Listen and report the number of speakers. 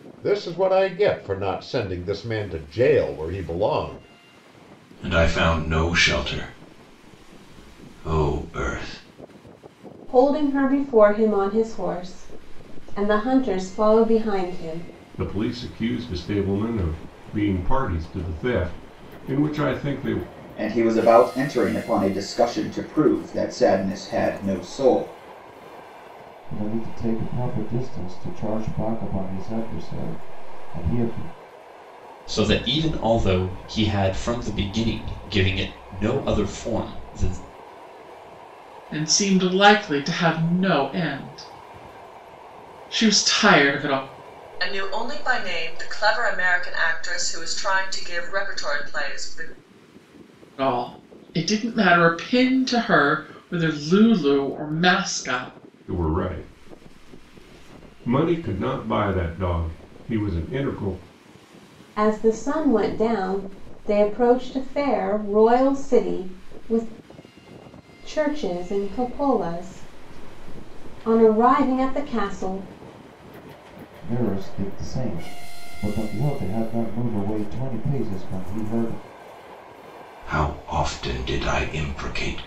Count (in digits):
9